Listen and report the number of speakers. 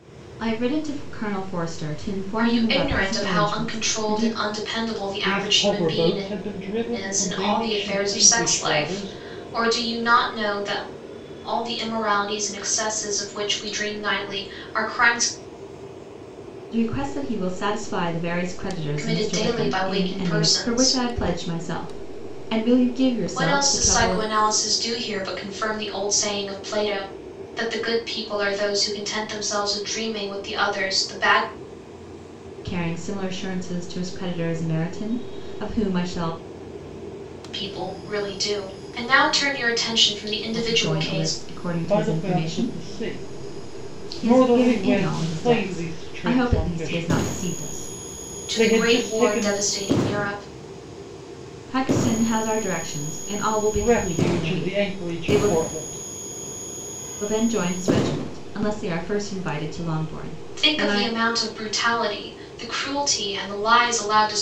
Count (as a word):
three